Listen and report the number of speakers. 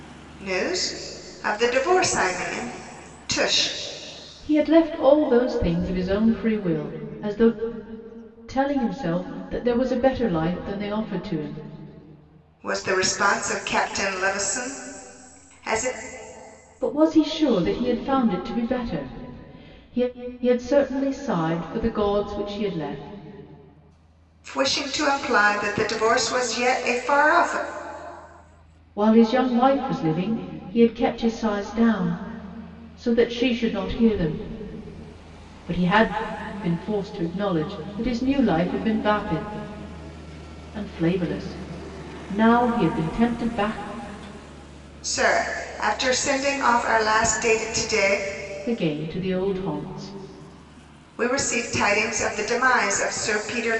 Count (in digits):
2